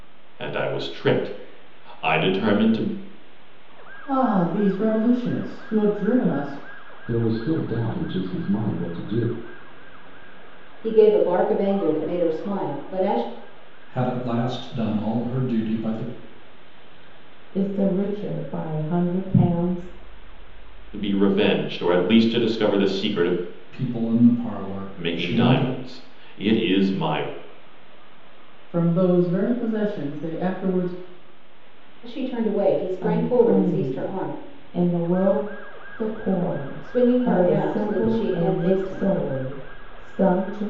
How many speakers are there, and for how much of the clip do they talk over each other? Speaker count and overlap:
six, about 11%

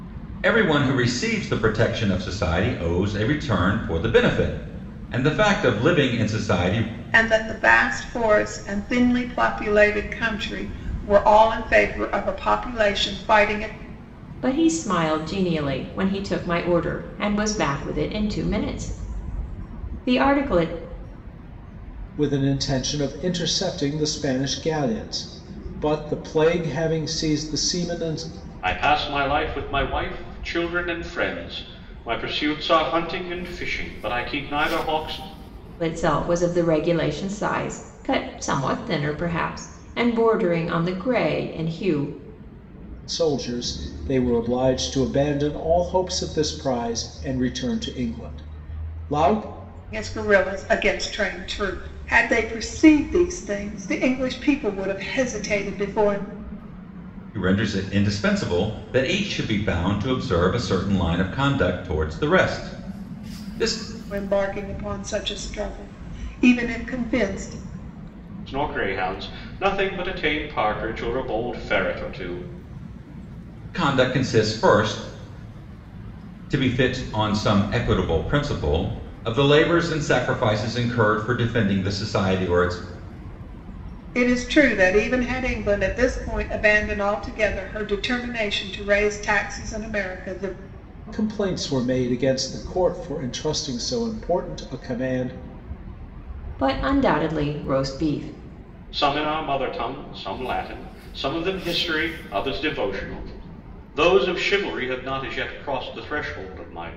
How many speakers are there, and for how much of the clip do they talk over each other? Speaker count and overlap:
five, no overlap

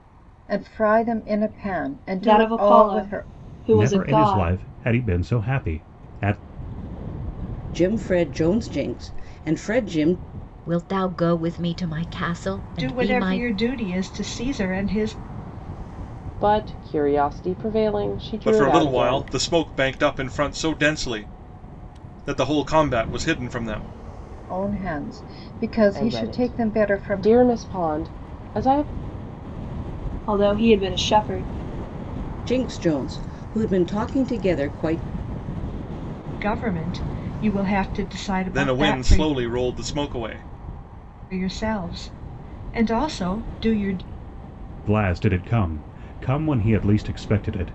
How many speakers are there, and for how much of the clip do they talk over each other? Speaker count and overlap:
eight, about 12%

